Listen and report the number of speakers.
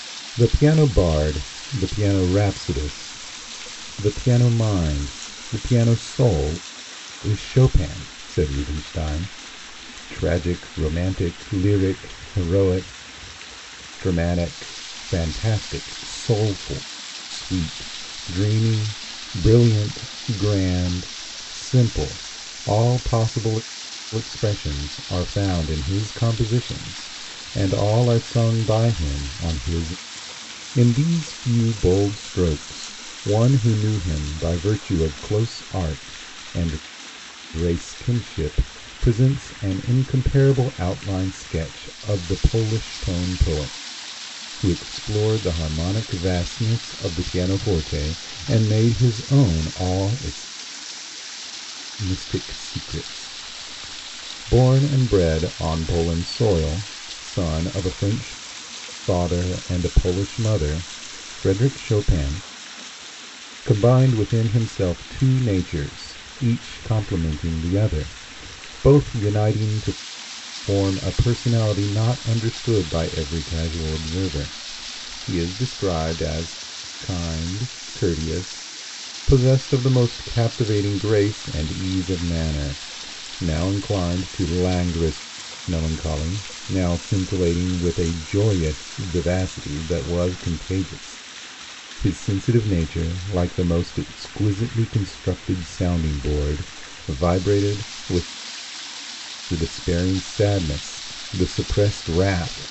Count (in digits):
1